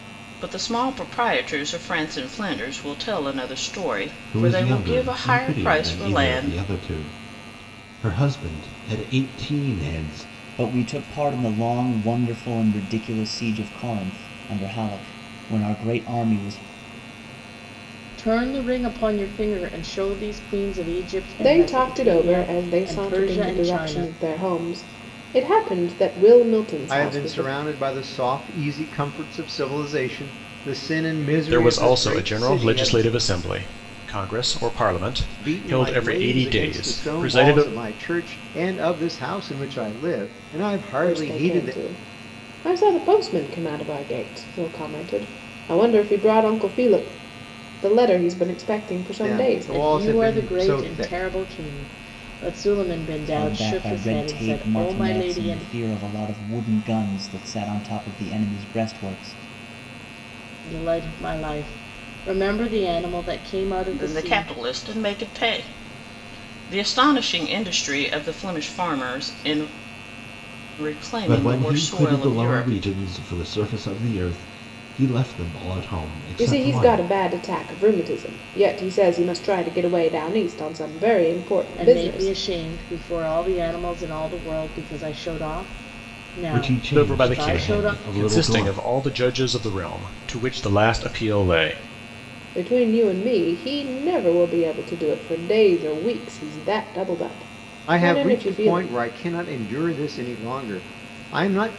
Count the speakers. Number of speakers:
seven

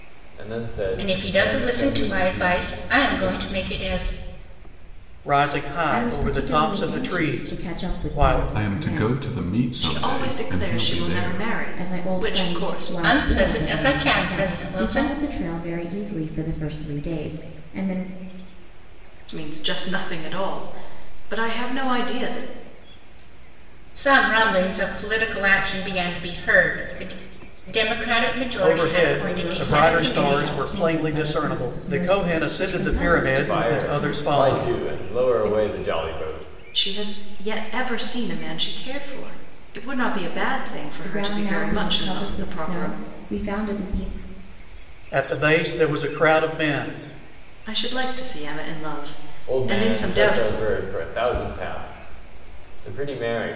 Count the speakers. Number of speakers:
six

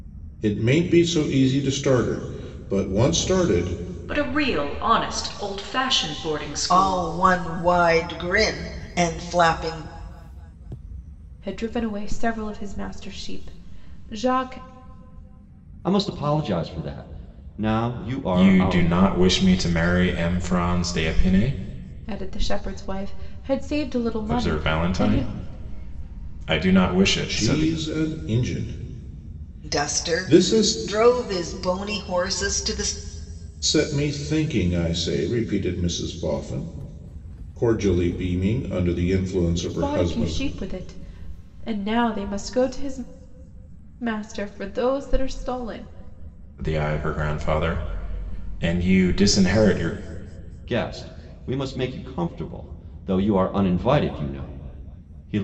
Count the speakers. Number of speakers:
six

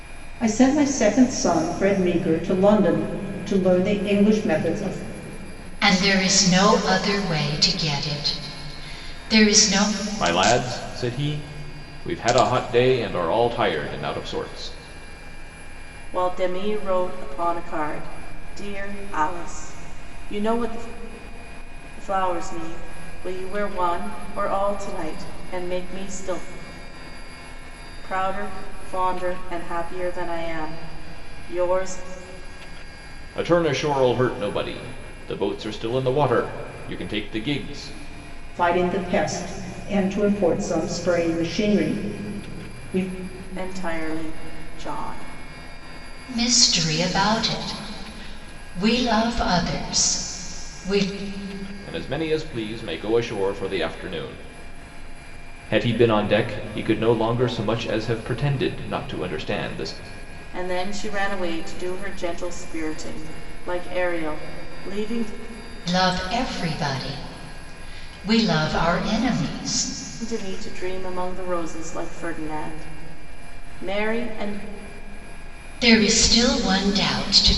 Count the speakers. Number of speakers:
four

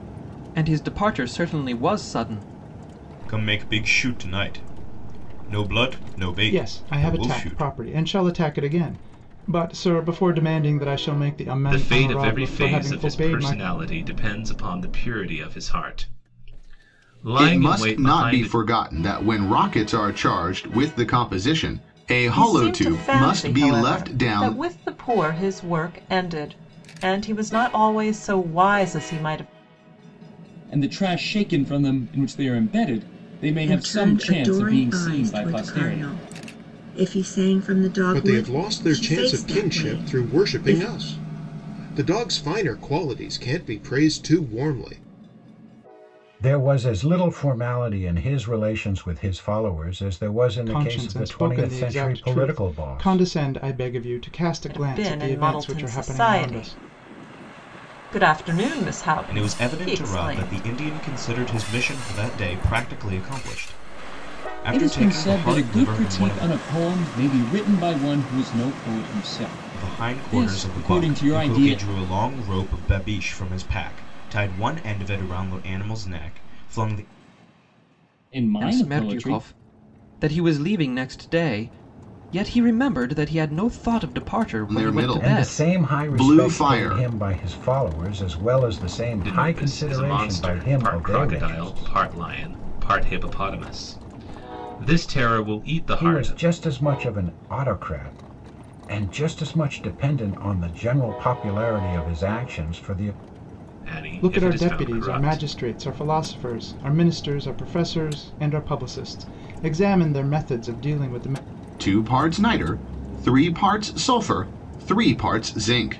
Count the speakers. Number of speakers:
ten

